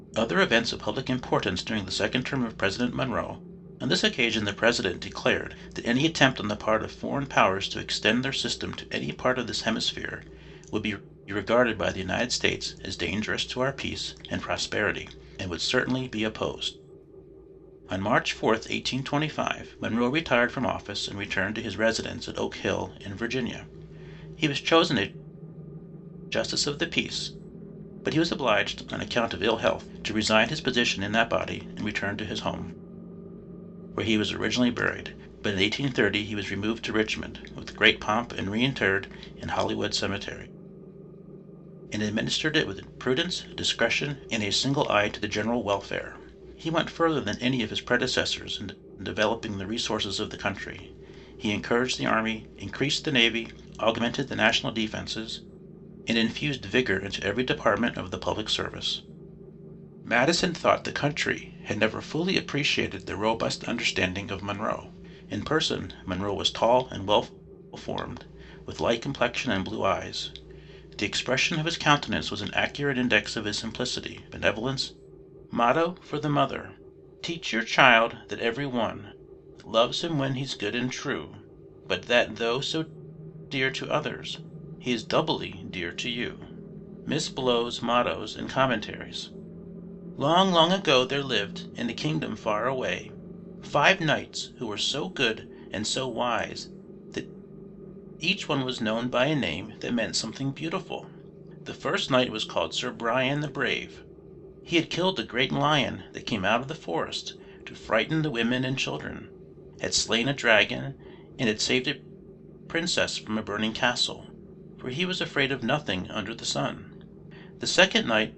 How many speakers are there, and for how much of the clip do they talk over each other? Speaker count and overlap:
one, no overlap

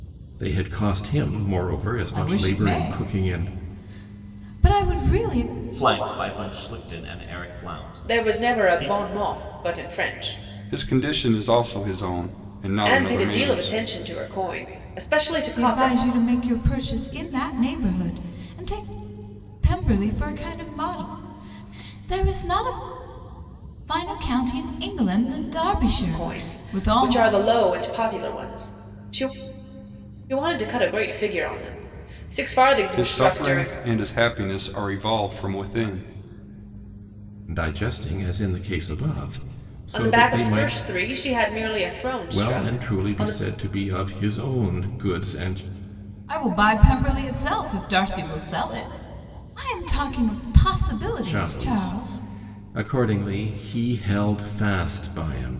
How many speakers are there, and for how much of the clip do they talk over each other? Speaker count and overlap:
five, about 16%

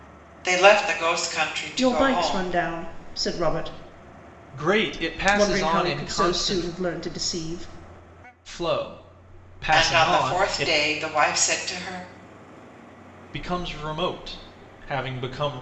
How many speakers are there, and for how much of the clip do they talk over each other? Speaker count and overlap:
three, about 21%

